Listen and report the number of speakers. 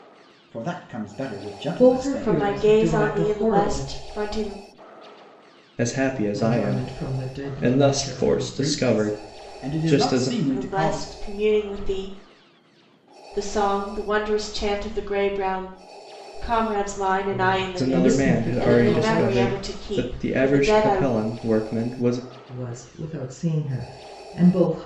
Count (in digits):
4